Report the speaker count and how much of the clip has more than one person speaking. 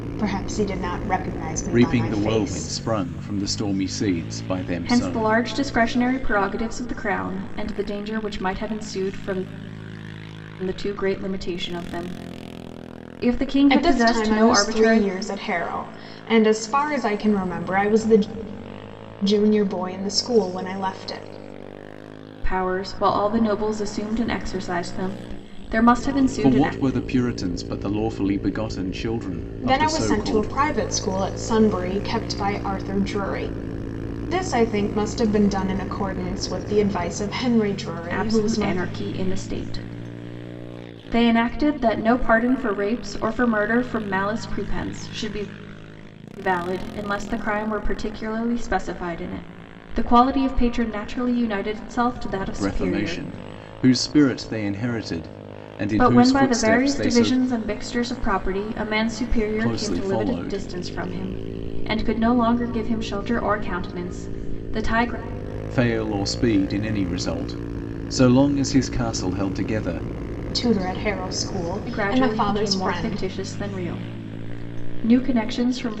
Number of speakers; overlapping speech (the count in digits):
3, about 13%